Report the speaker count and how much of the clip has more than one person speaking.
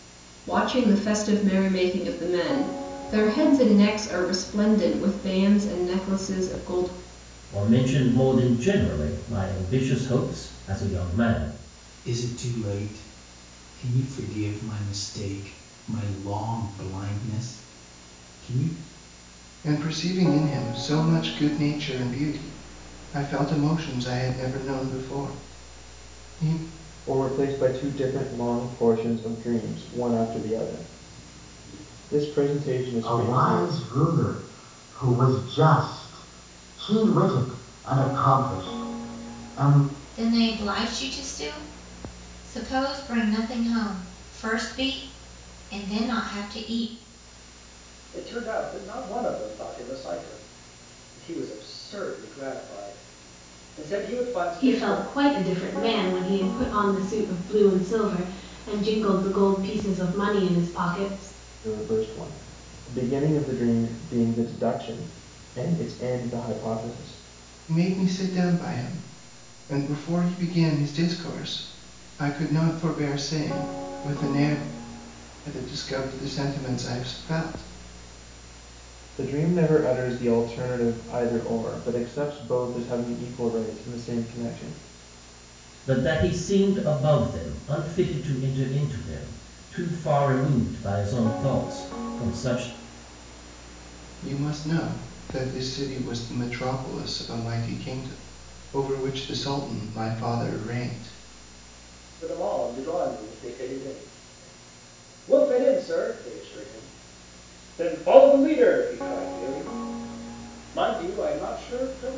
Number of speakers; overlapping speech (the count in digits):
9, about 1%